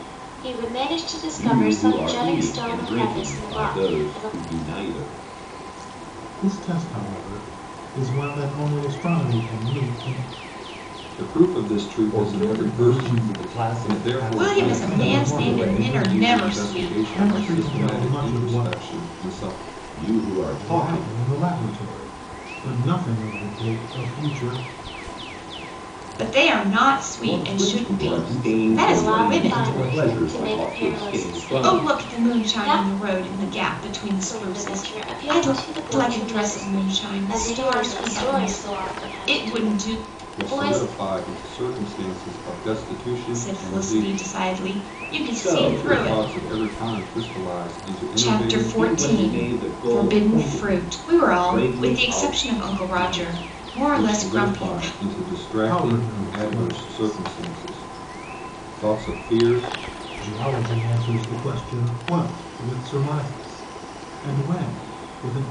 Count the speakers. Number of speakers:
6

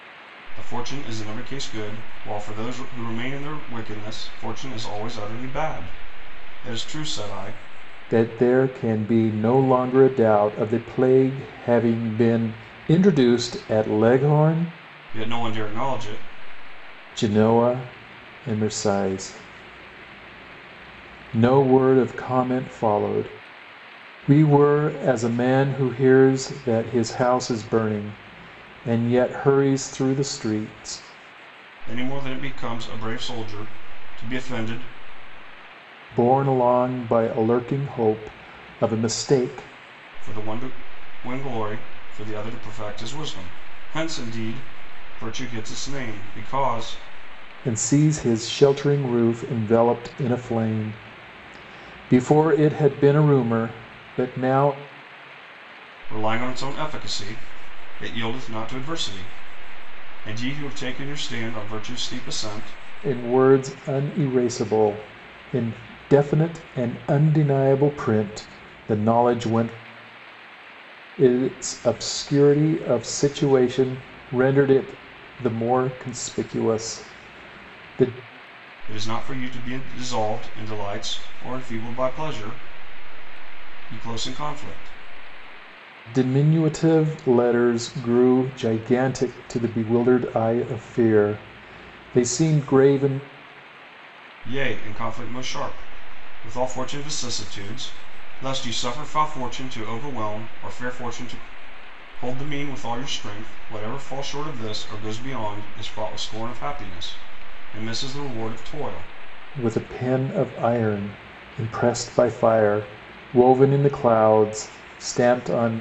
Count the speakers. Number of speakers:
2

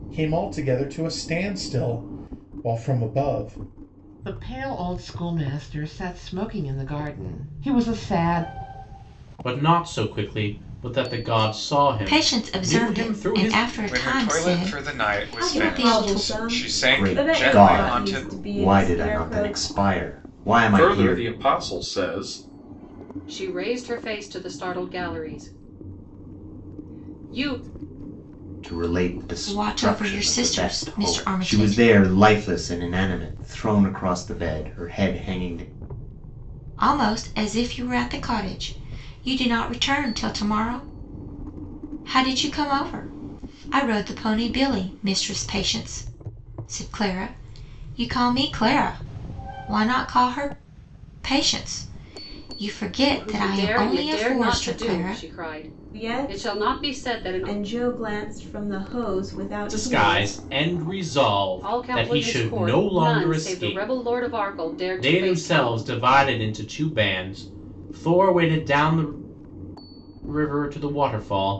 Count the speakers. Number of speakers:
9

